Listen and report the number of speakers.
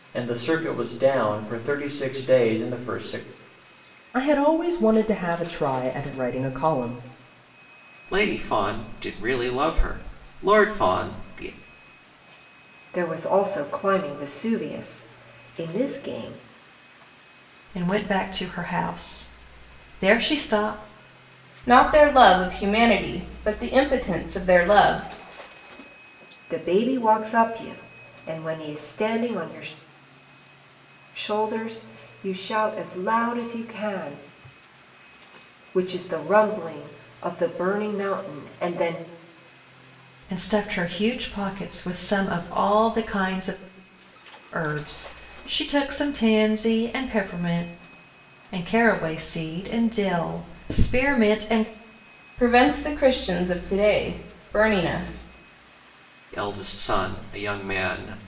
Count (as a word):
six